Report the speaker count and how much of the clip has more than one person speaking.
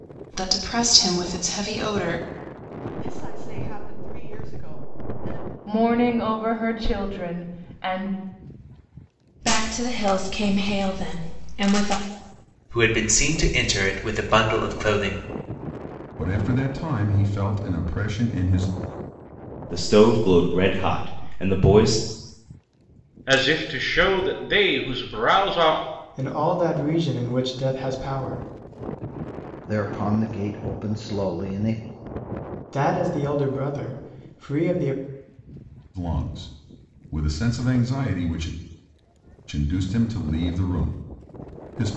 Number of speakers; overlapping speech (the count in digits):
10, no overlap